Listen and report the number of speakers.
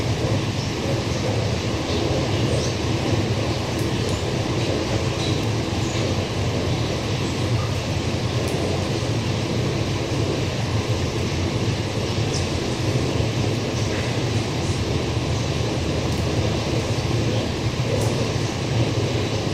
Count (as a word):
zero